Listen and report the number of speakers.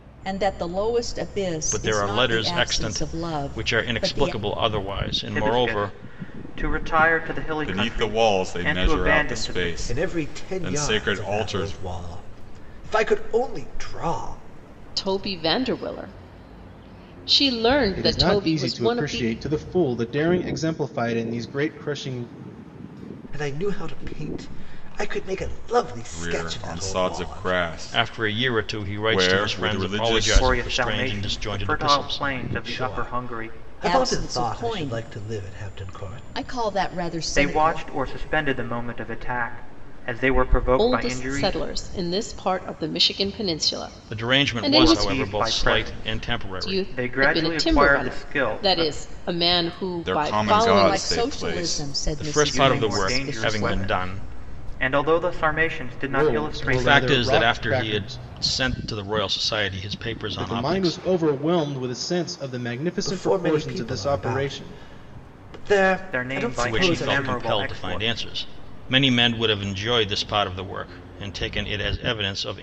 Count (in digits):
7